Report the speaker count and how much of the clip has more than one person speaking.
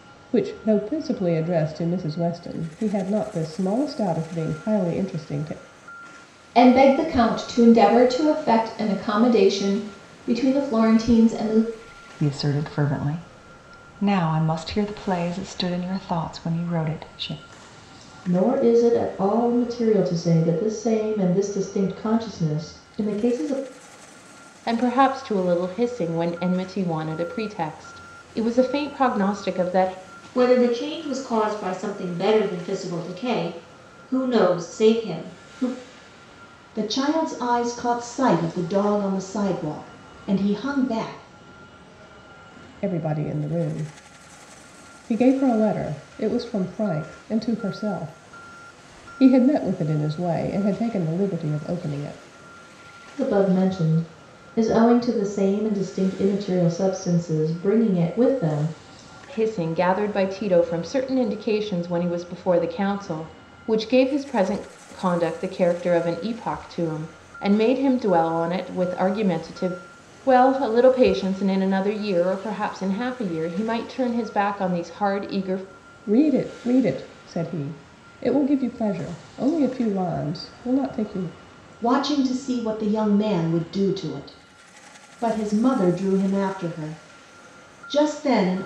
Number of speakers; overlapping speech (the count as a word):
seven, no overlap